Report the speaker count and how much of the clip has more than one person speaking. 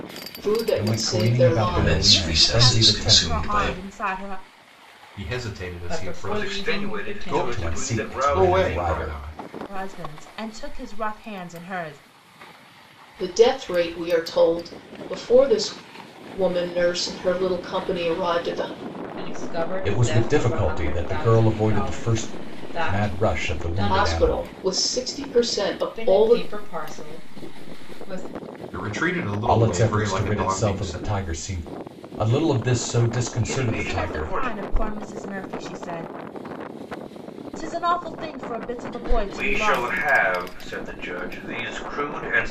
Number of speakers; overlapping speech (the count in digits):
7, about 35%